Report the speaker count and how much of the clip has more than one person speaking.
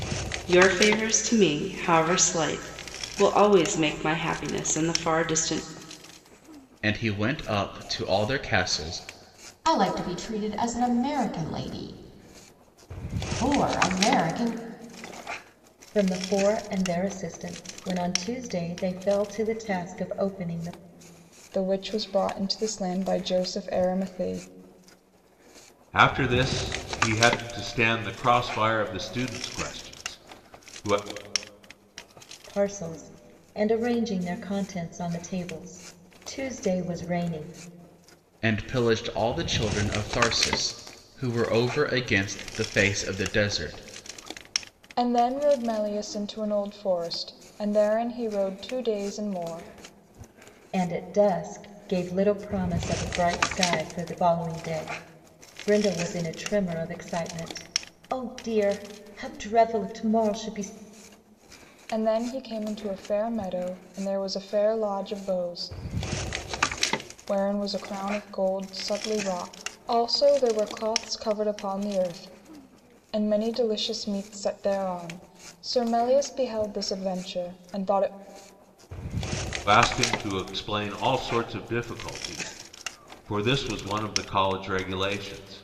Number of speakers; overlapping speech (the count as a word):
six, no overlap